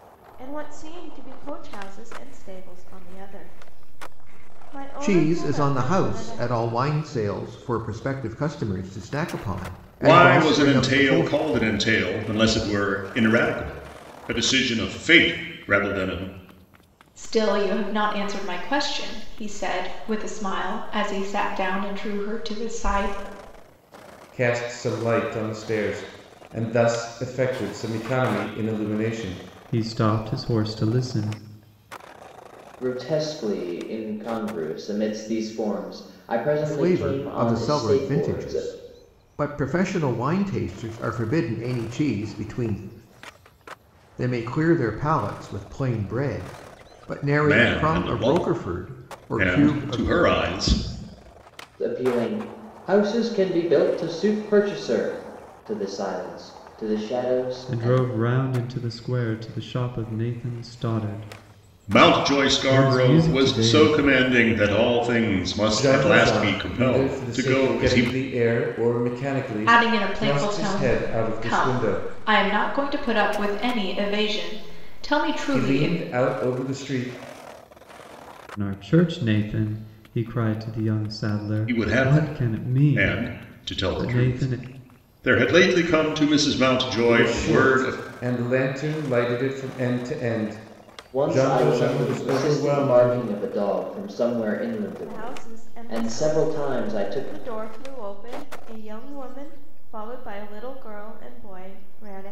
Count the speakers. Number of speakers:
7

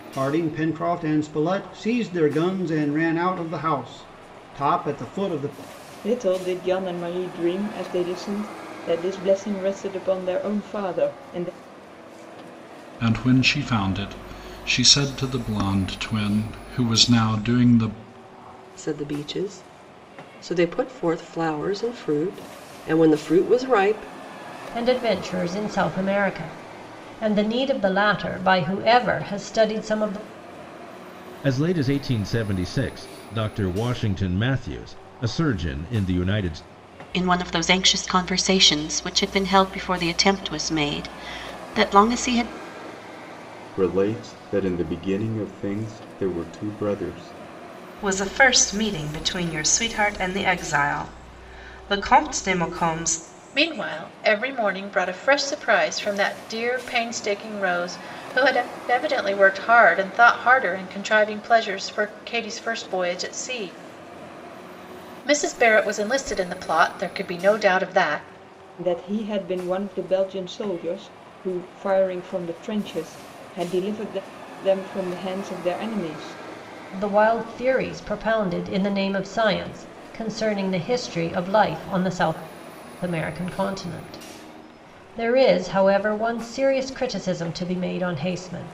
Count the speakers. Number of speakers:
10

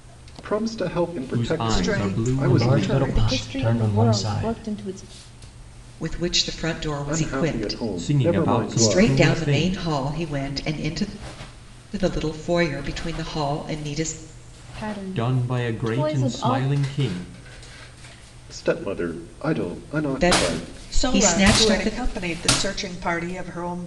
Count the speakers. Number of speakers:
6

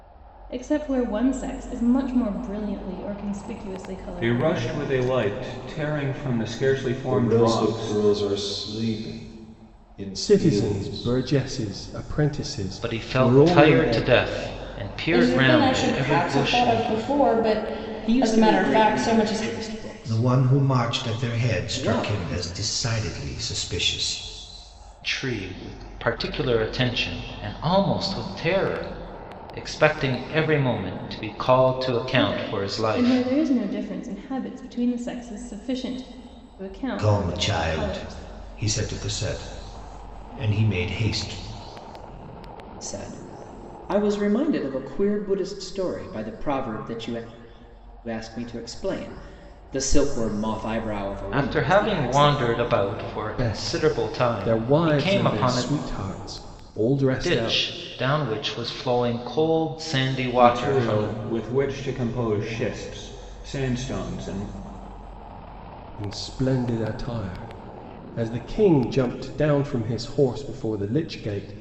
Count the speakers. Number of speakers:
8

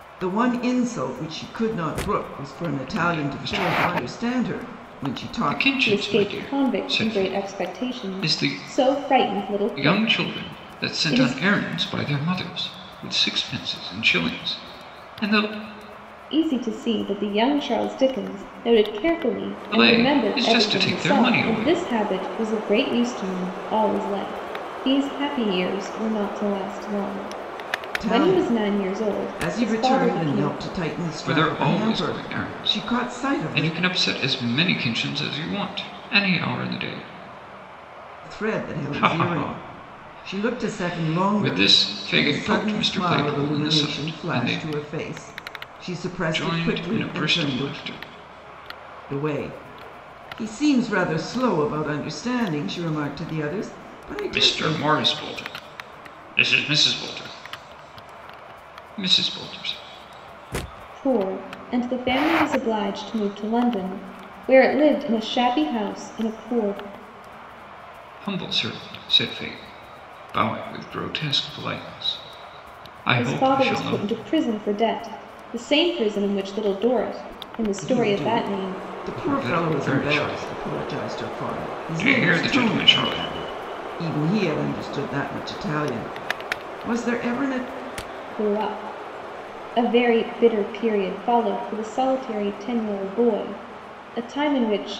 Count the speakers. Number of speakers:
3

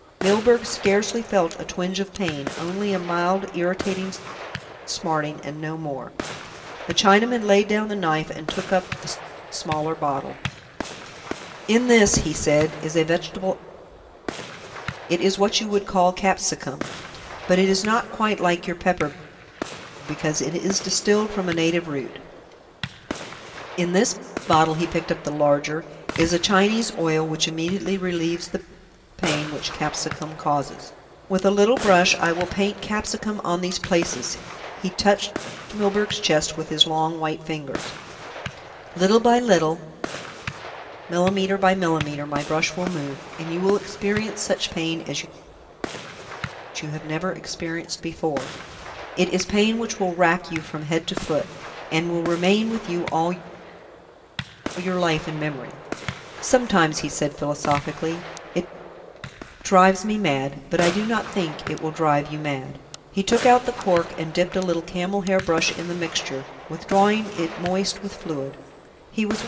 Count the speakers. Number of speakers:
1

